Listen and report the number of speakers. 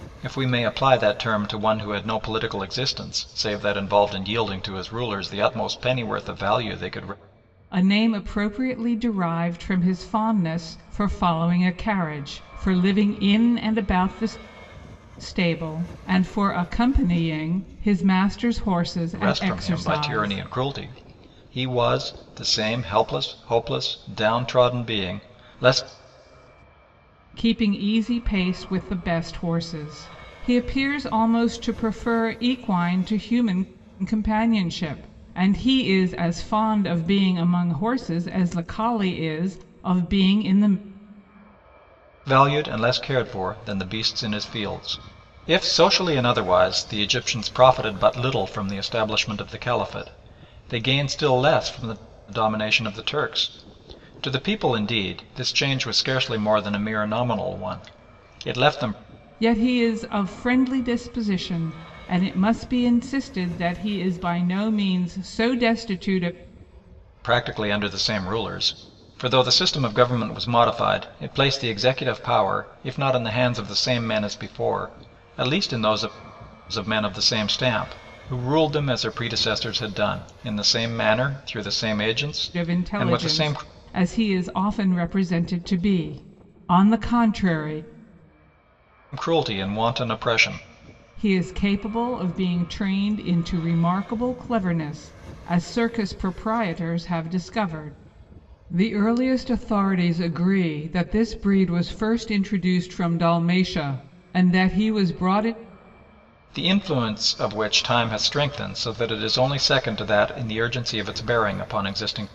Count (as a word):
two